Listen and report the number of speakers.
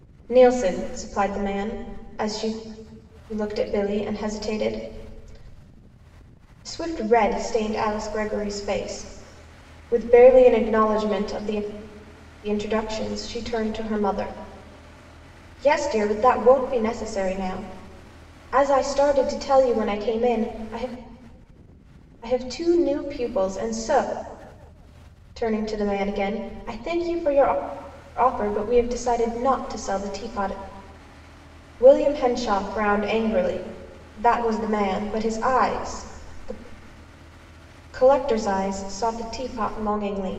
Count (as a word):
one